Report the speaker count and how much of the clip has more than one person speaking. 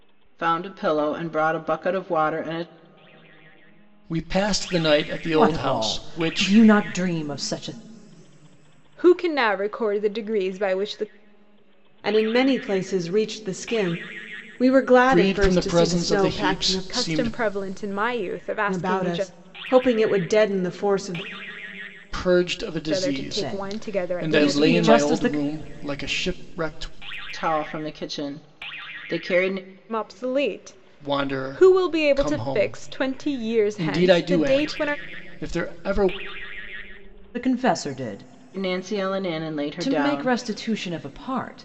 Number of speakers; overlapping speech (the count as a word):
five, about 28%